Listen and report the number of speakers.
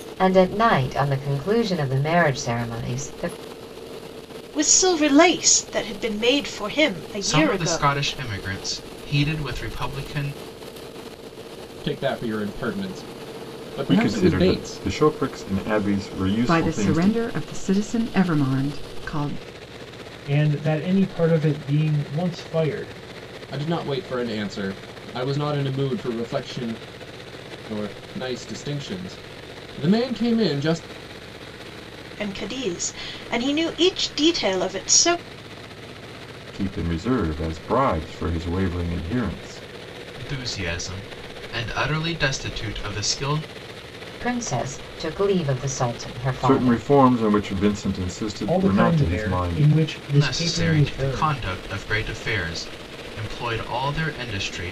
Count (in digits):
7